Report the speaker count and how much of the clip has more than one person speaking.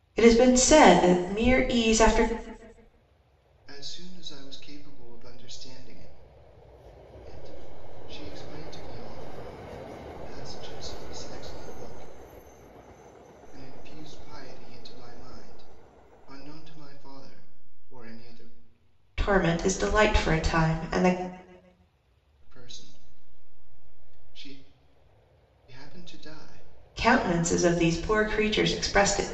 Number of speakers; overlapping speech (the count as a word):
two, no overlap